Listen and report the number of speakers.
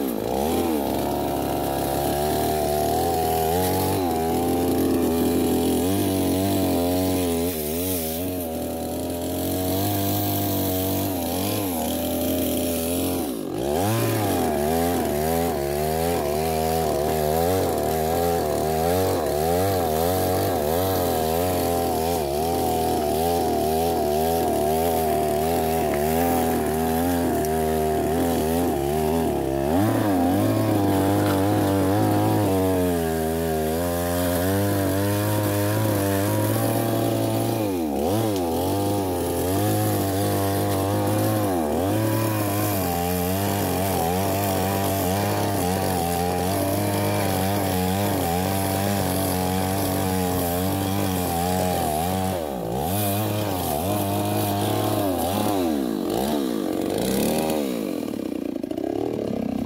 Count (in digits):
0